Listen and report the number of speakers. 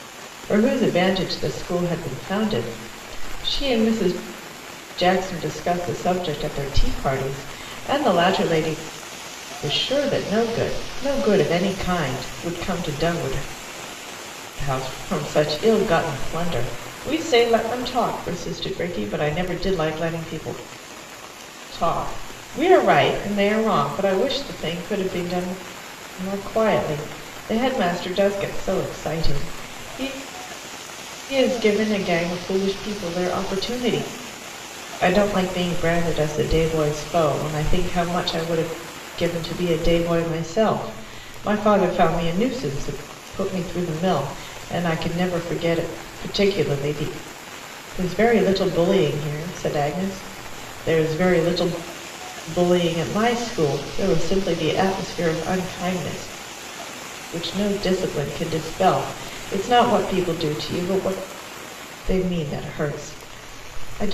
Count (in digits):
1